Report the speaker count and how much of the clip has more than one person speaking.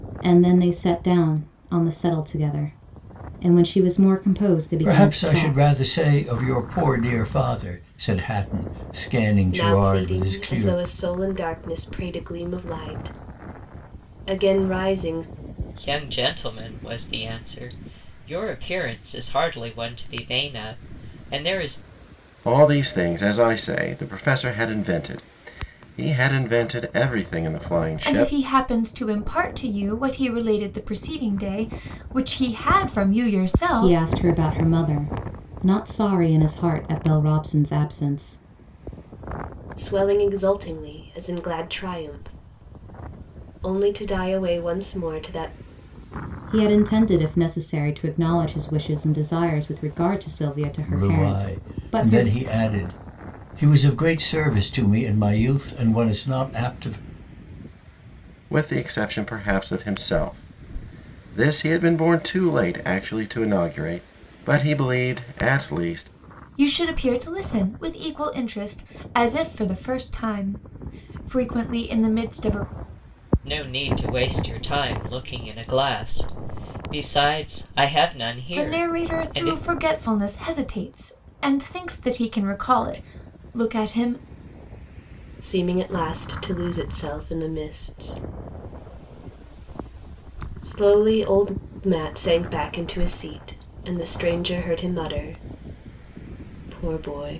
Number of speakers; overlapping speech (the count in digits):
6, about 6%